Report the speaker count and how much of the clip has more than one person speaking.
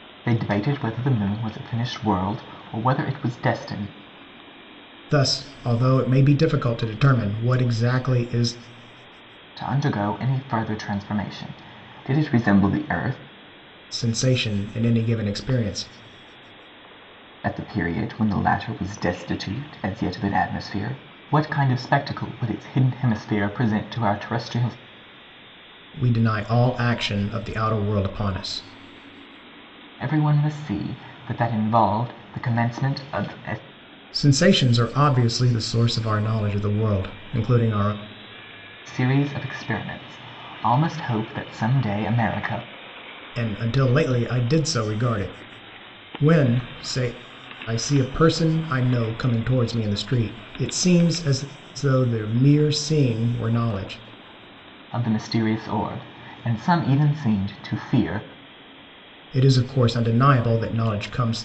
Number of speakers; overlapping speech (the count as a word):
two, no overlap